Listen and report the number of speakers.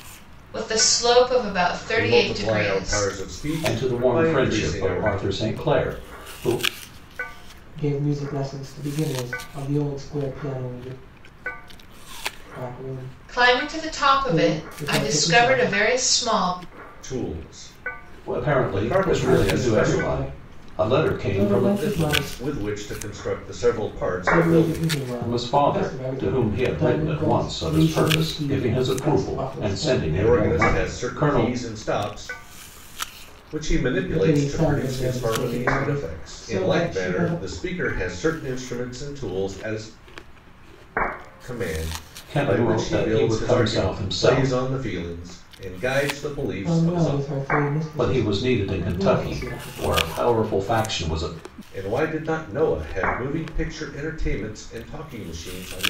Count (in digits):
4